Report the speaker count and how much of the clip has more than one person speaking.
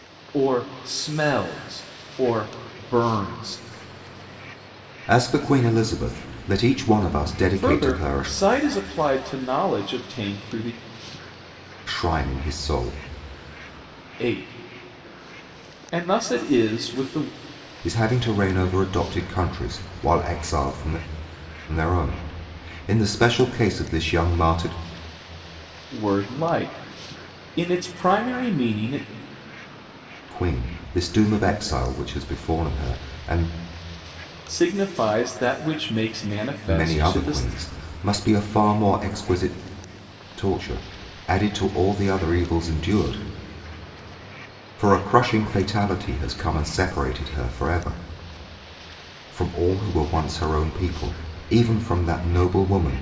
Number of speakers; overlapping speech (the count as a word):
two, about 3%